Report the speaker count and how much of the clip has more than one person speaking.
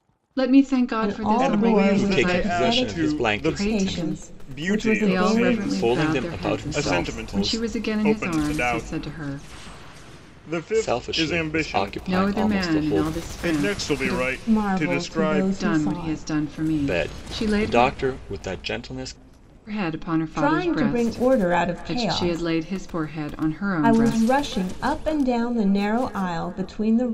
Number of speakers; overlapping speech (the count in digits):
4, about 62%